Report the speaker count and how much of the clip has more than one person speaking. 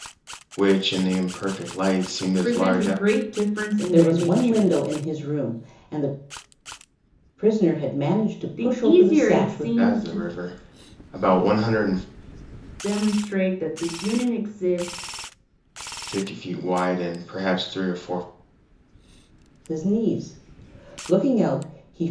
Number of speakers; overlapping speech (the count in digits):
3, about 15%